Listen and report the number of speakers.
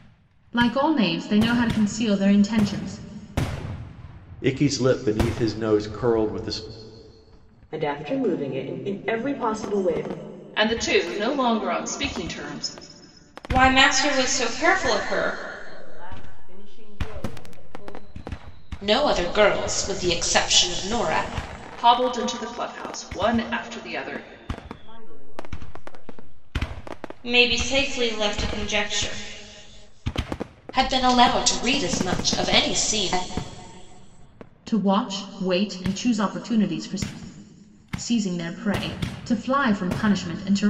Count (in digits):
7